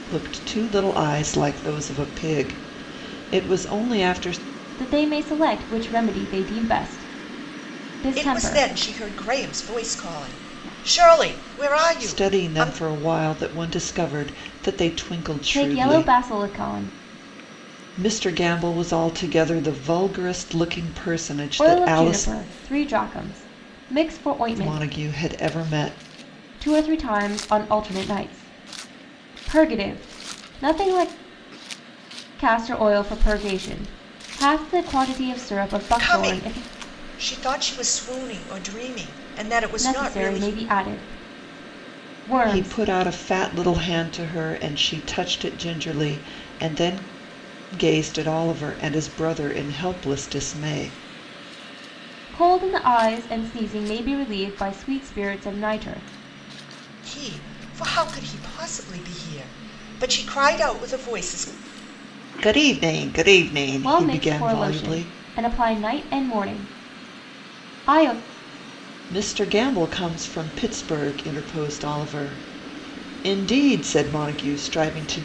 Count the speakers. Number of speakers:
3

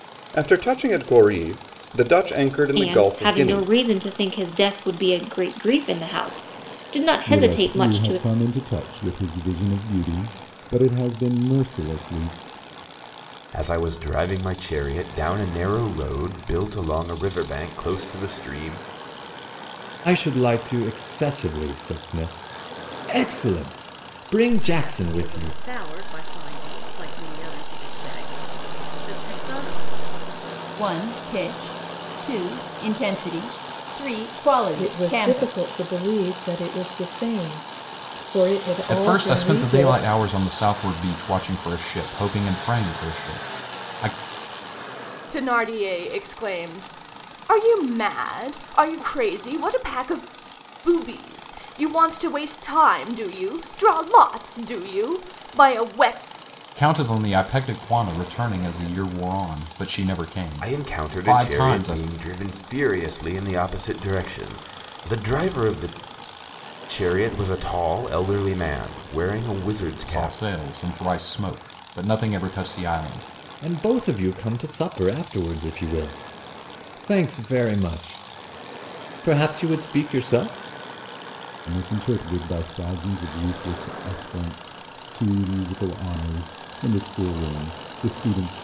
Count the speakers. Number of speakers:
10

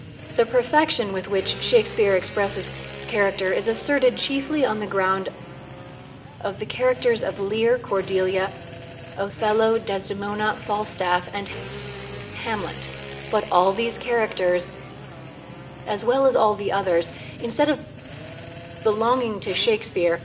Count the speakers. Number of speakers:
1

